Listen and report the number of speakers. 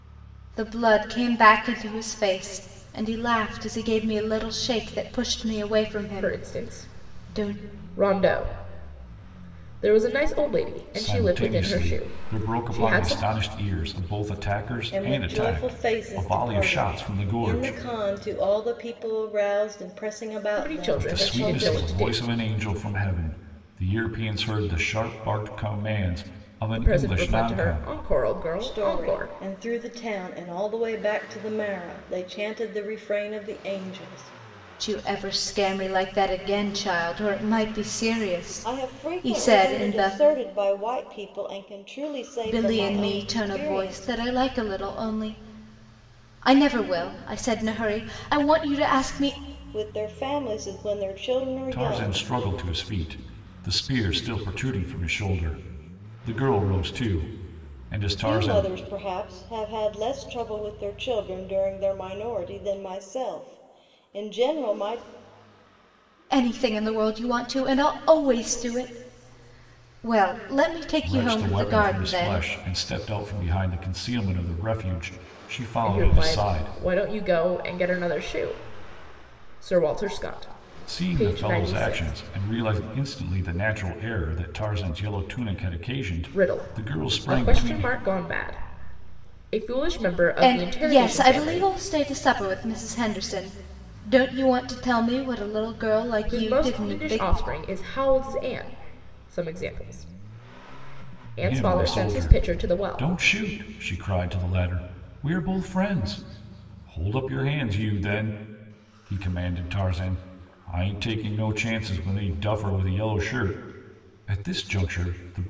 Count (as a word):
four